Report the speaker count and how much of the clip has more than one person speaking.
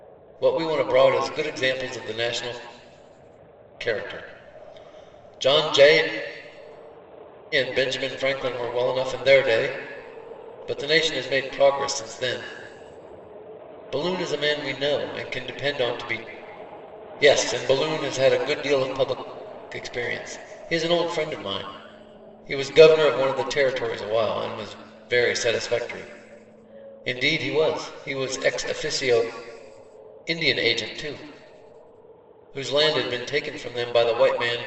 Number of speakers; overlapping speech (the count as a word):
one, no overlap